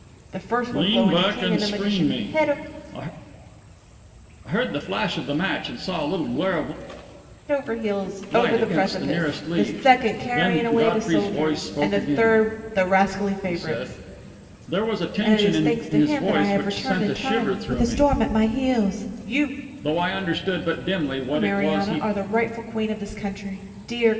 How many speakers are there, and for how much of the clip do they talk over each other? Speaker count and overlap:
2, about 41%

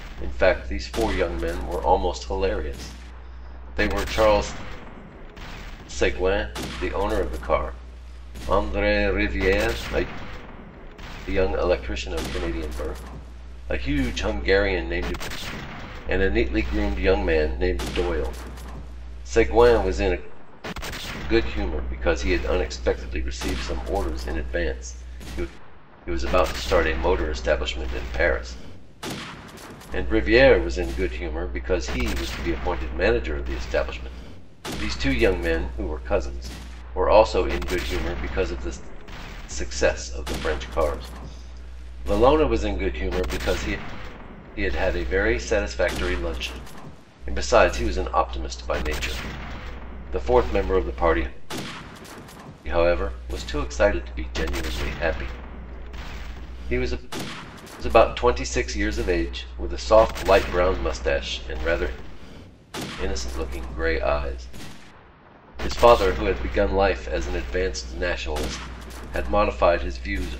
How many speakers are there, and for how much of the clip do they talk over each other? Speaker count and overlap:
1, no overlap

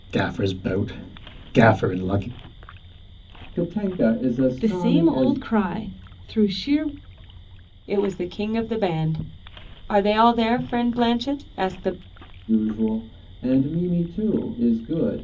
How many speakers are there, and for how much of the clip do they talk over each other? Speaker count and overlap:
4, about 6%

